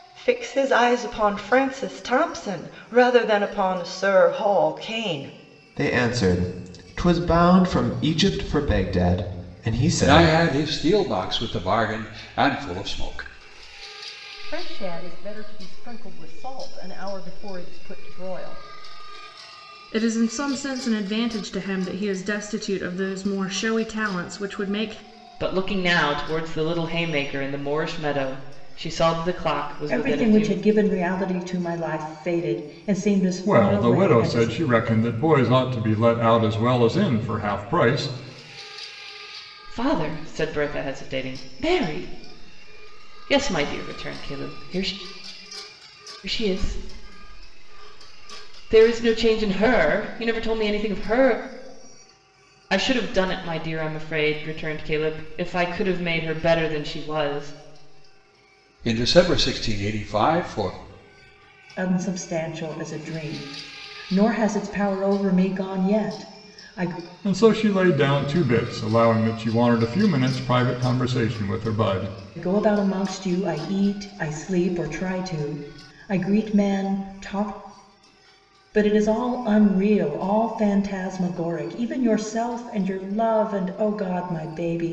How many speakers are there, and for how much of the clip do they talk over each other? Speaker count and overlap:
eight, about 3%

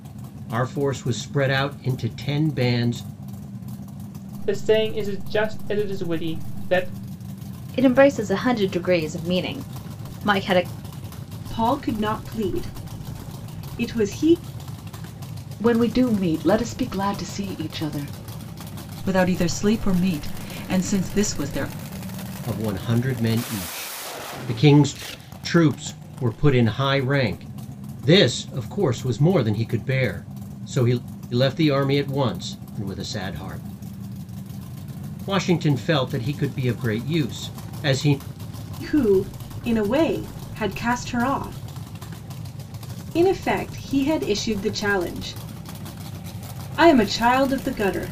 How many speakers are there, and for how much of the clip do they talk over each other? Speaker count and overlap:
six, no overlap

